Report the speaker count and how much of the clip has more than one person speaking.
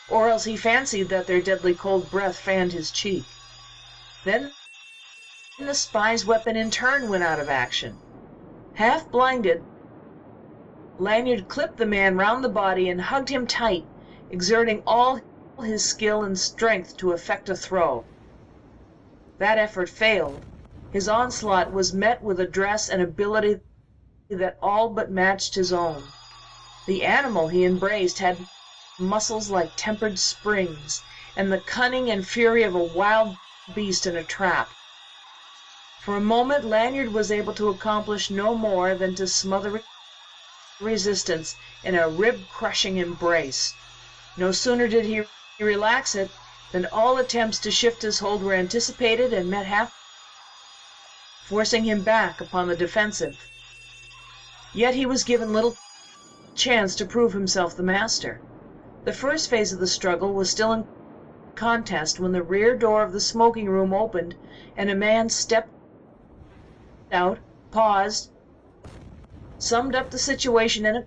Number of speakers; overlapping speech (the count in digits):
1, no overlap